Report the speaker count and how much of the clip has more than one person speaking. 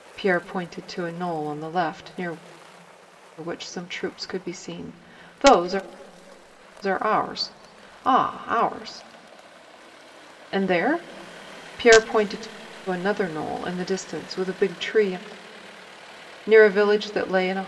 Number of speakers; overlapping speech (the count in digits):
1, no overlap